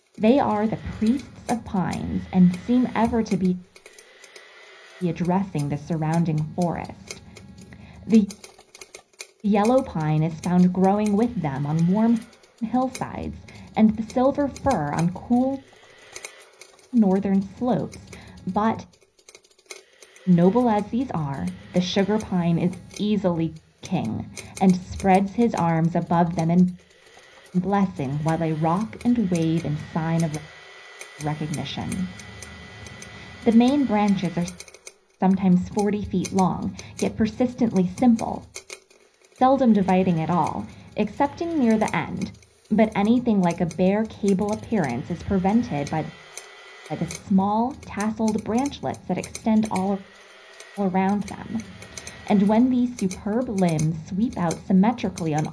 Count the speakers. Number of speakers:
1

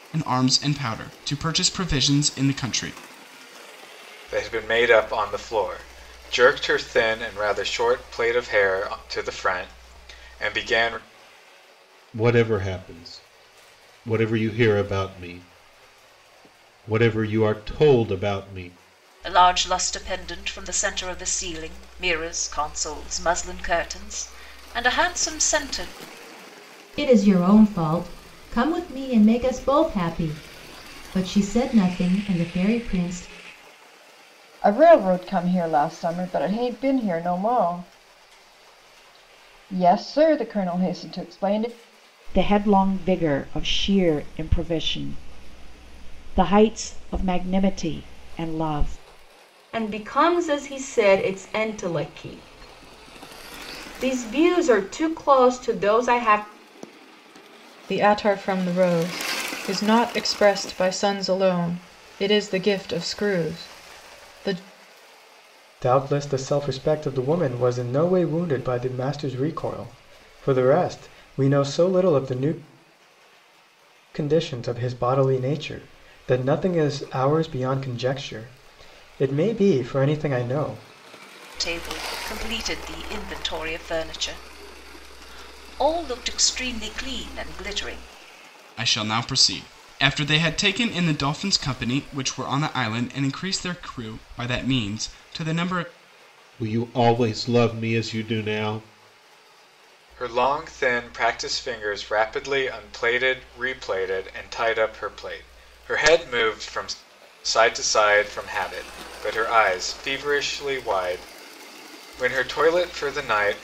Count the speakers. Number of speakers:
10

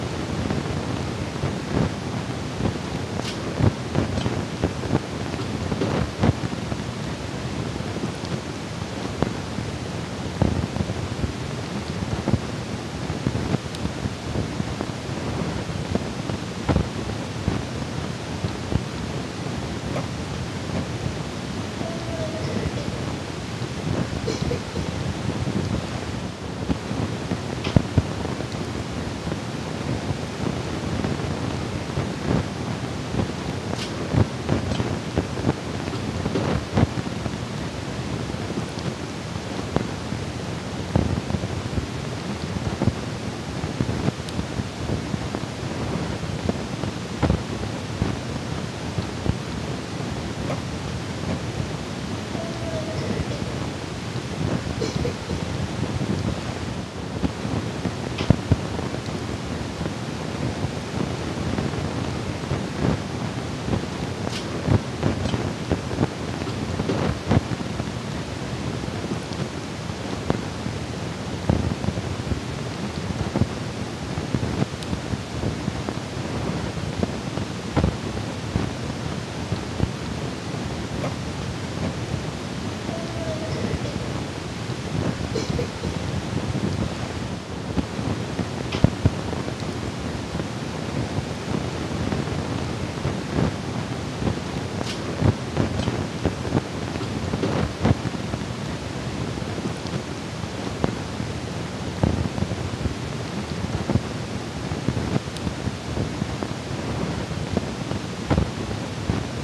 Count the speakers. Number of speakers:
0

